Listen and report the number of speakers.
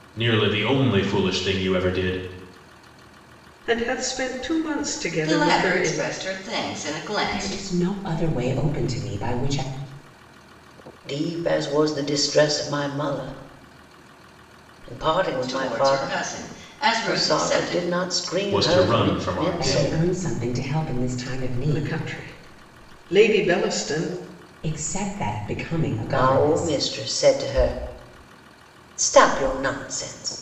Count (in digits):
5